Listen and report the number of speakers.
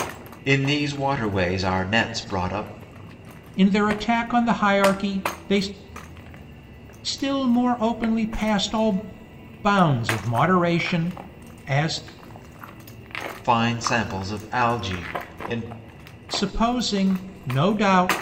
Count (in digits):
2